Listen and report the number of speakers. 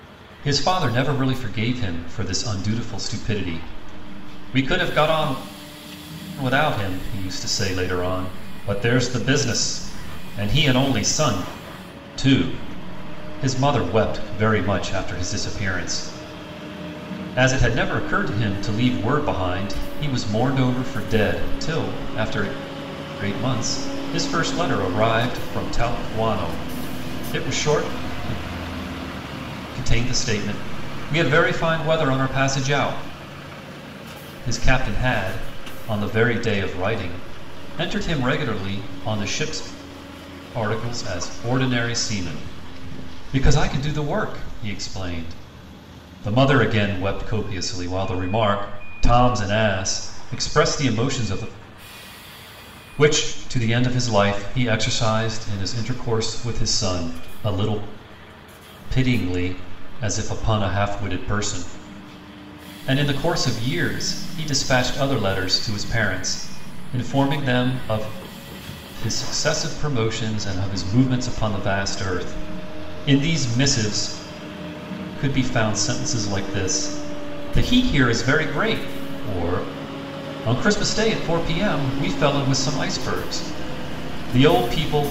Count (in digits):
1